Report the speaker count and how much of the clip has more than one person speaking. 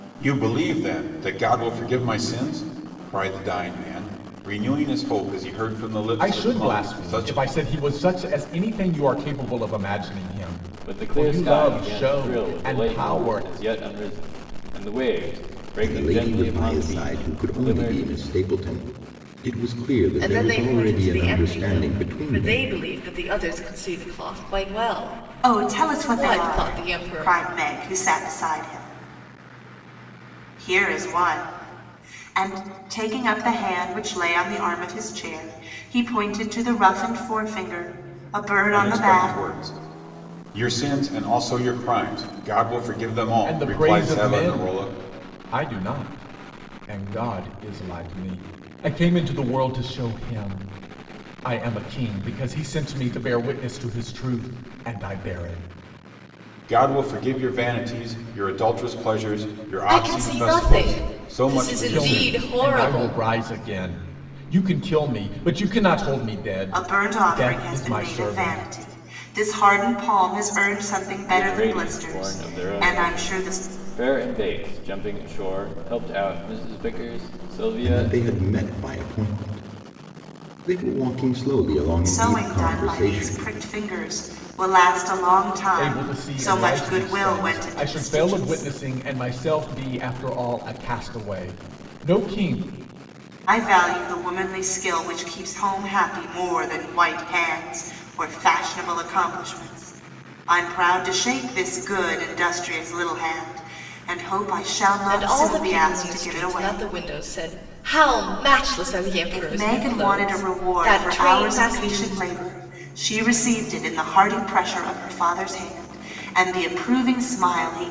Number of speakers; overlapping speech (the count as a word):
six, about 26%